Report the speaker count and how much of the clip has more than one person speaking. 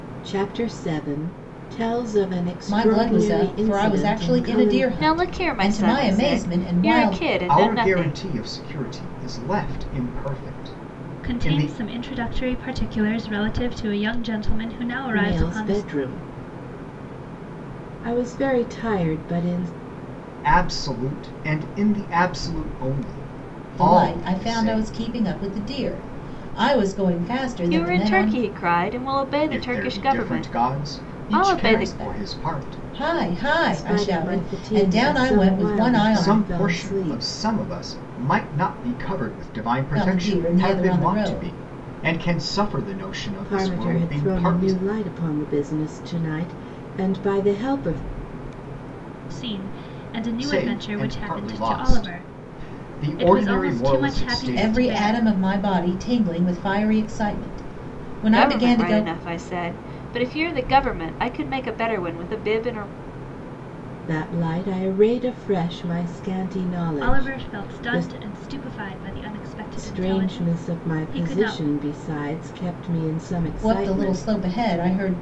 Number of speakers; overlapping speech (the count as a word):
five, about 36%